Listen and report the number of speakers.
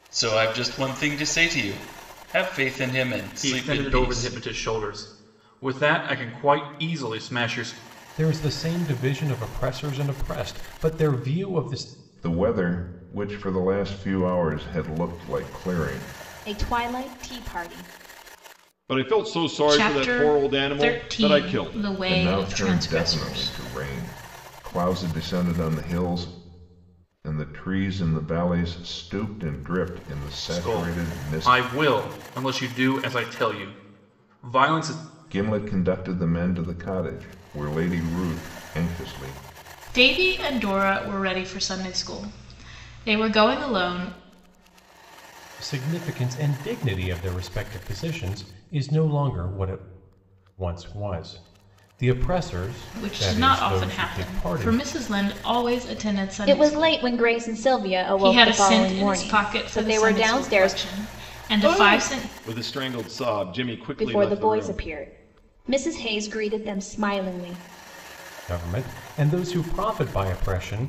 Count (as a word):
seven